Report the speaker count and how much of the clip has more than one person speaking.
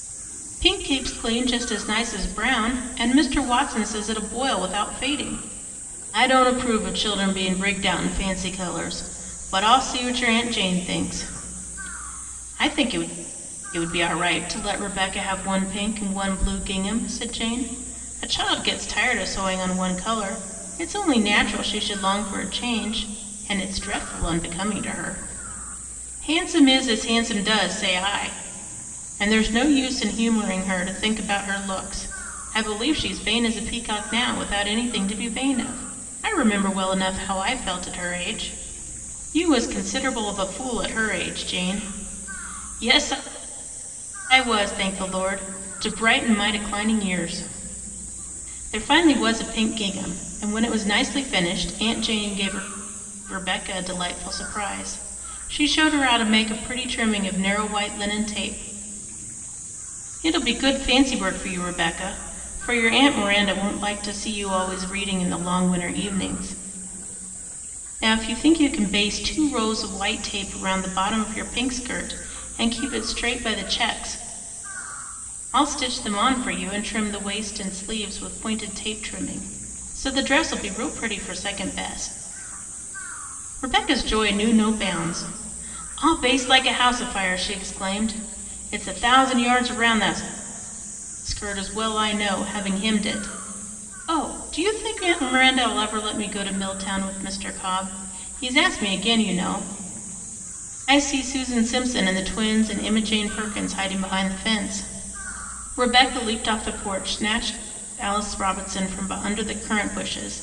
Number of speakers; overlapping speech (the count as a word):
one, no overlap